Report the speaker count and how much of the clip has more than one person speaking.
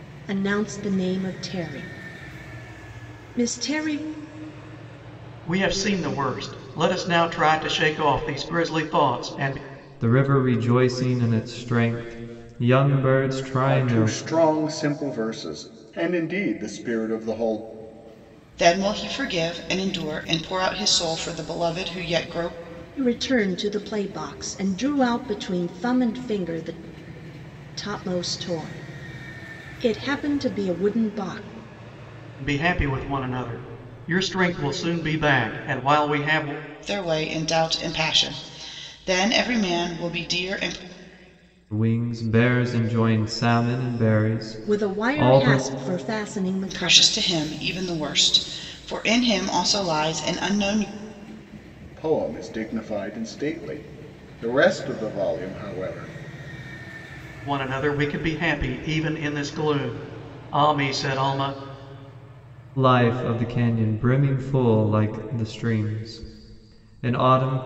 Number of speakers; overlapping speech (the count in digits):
5, about 3%